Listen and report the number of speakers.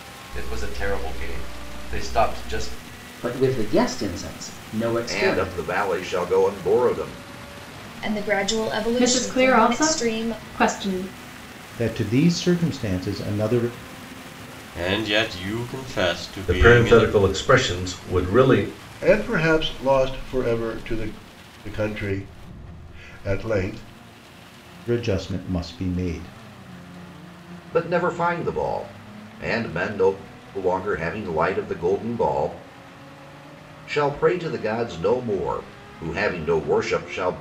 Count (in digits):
9